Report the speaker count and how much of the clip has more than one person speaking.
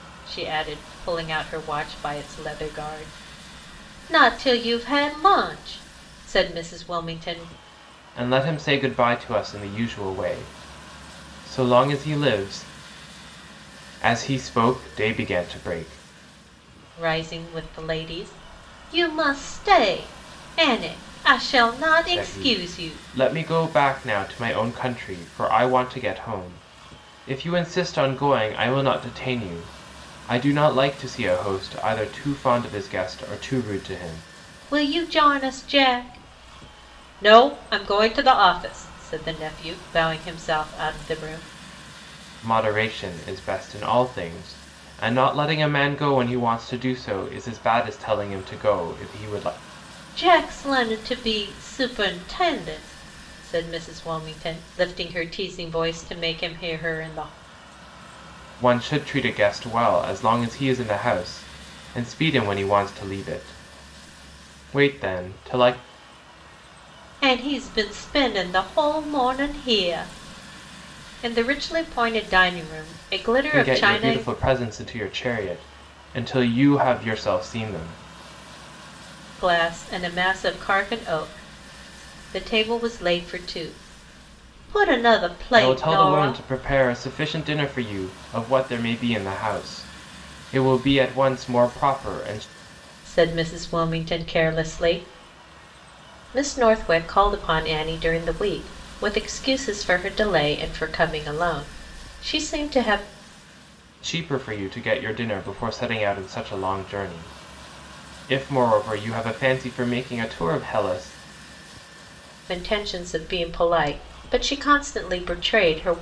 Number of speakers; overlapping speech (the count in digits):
2, about 2%